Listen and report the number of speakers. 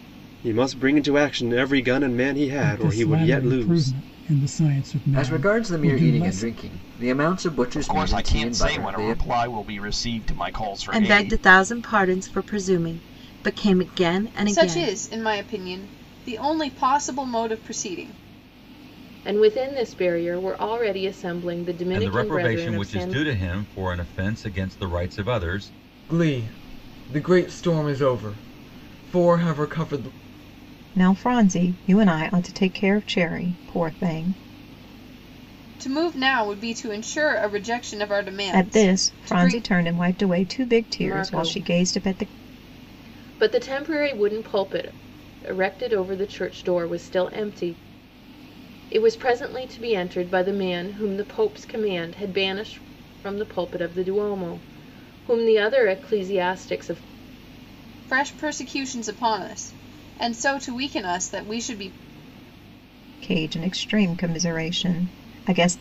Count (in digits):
10